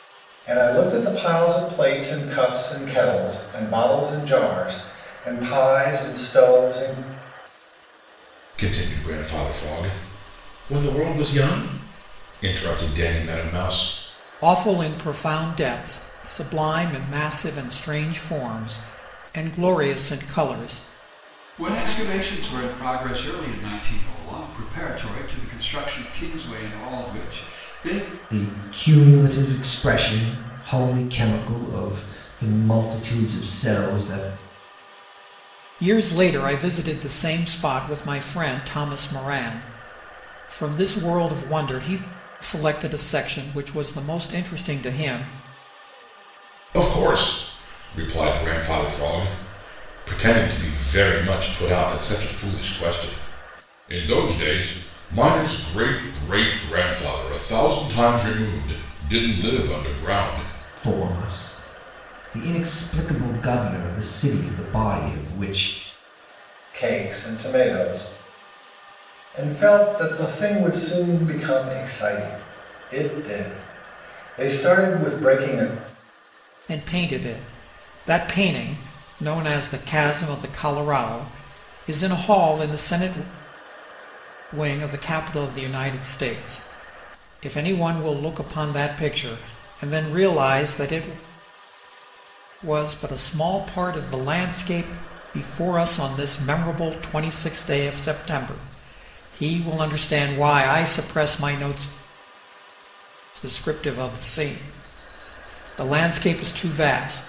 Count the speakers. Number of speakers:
five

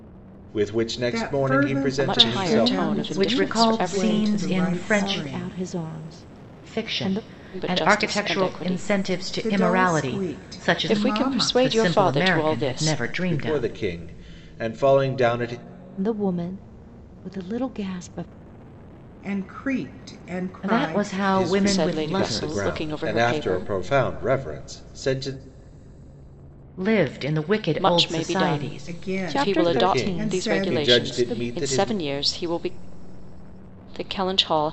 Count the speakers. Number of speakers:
five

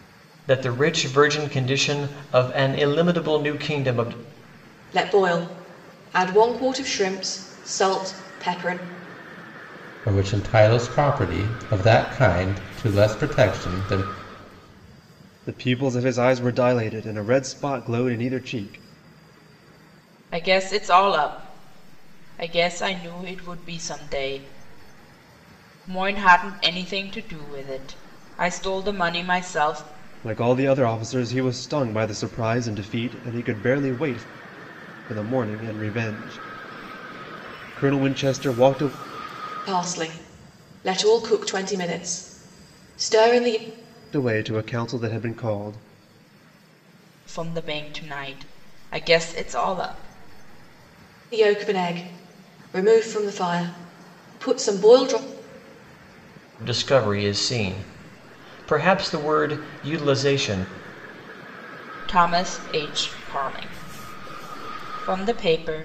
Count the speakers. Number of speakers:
five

